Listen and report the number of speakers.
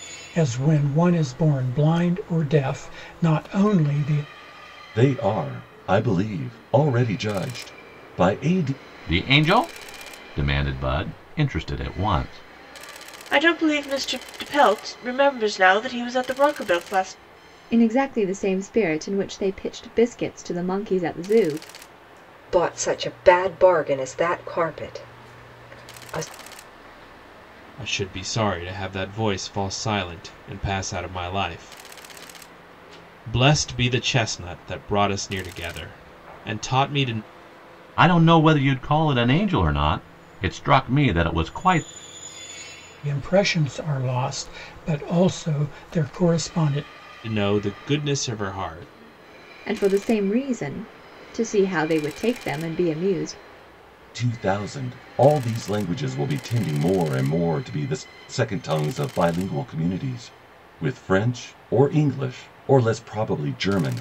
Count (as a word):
seven